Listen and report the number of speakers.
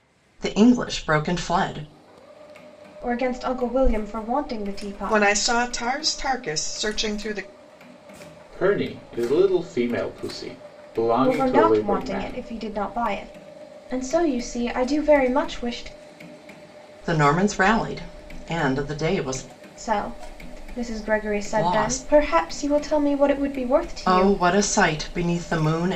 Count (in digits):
4